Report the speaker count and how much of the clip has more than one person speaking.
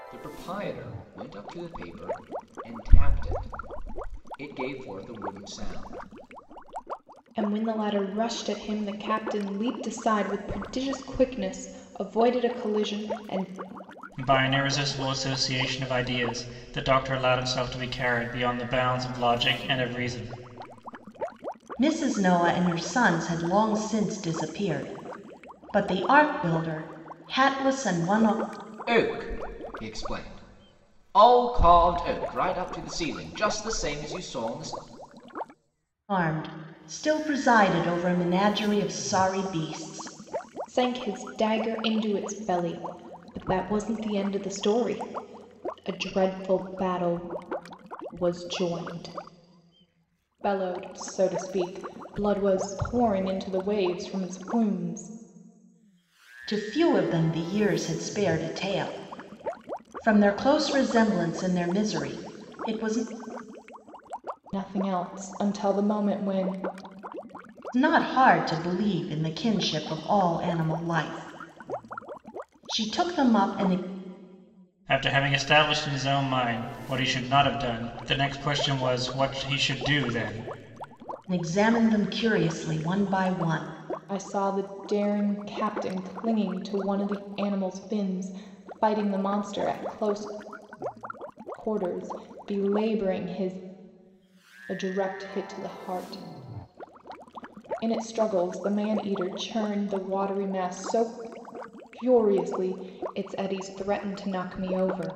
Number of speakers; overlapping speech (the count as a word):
four, no overlap